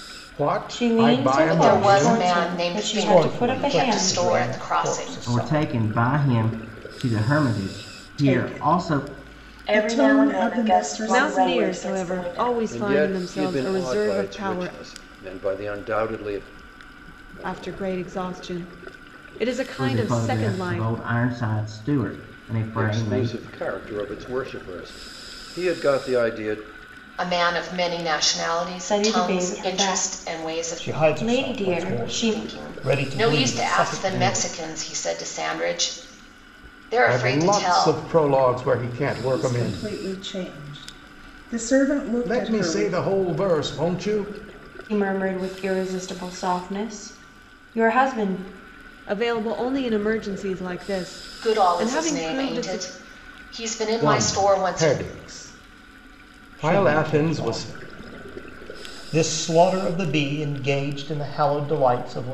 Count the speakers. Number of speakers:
nine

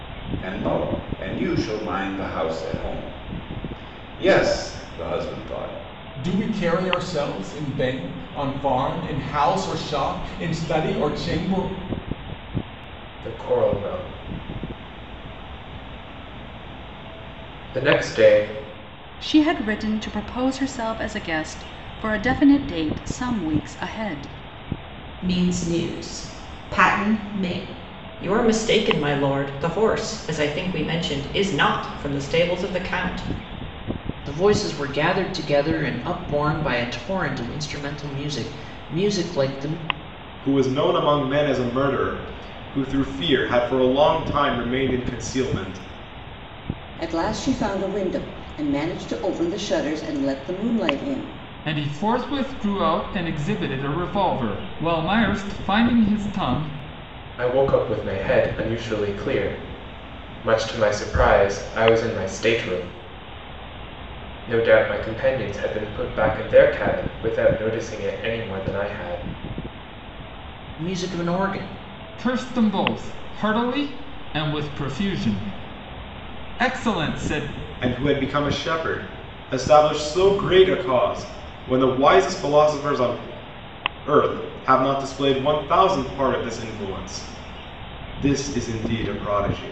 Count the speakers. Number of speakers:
ten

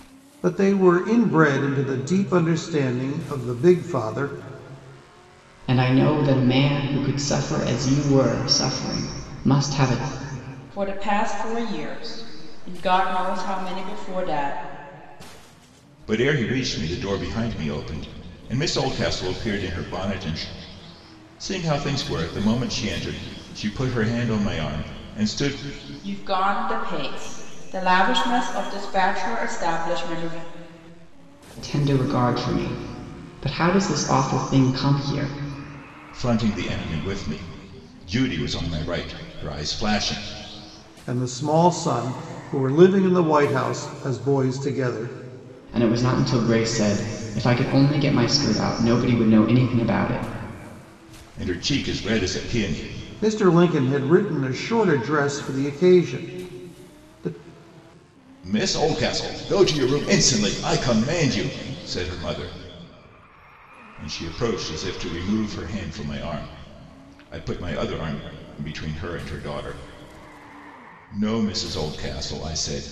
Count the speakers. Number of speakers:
four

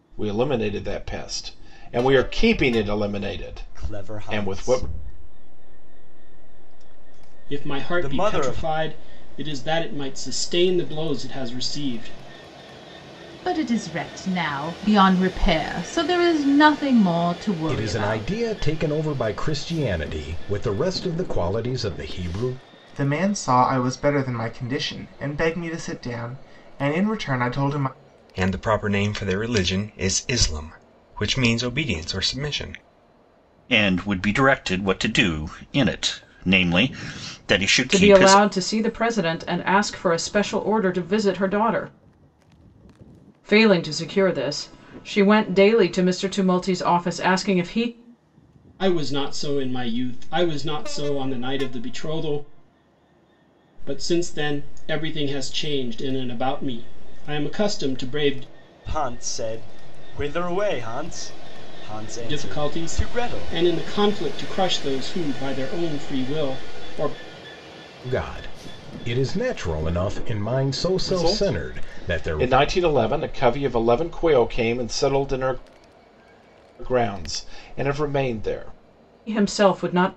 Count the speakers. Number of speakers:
nine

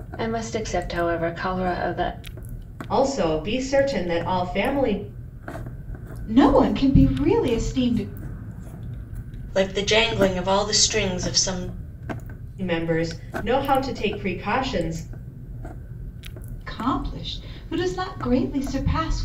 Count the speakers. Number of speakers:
four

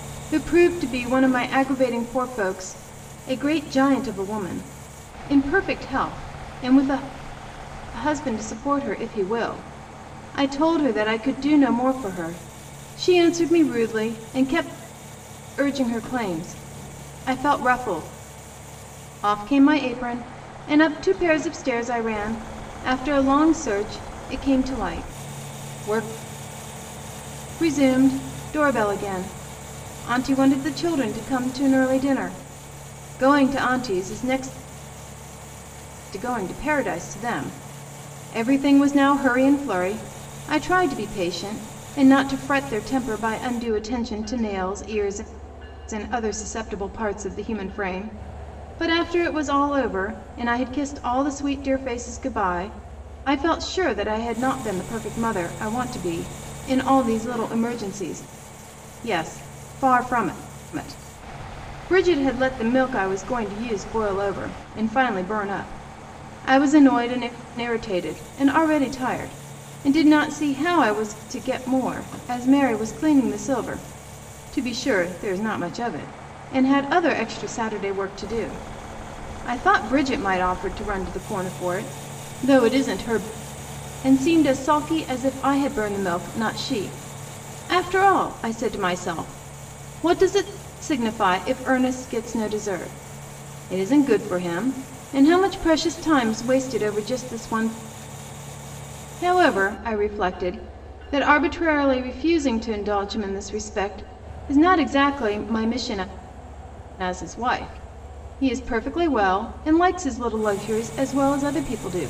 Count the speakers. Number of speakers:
one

